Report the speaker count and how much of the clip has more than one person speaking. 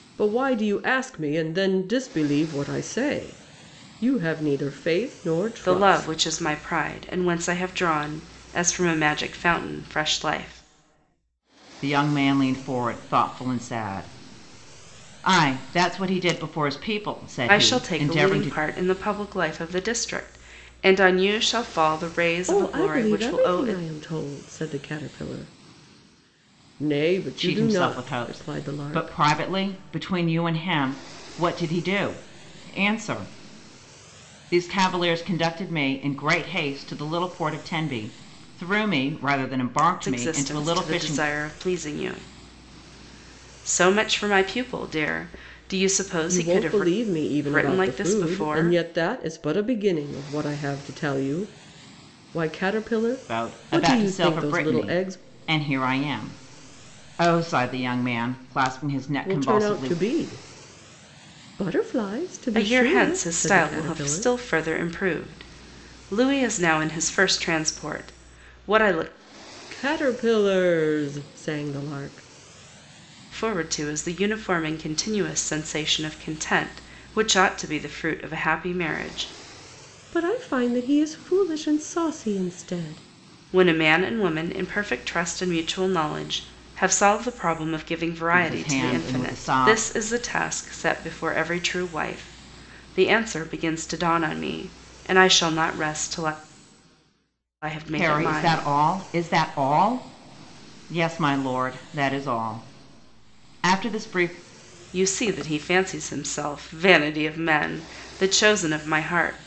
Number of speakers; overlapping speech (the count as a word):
three, about 14%